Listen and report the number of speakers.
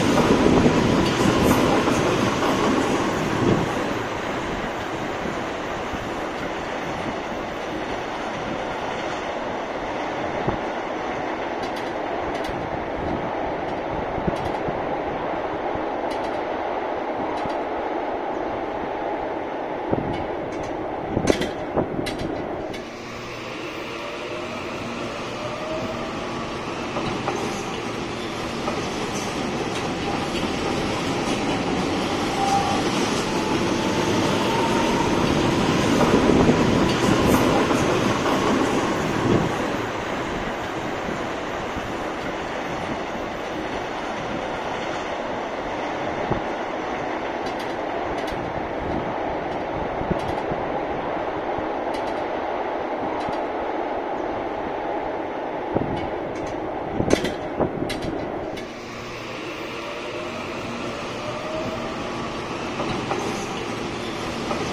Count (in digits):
0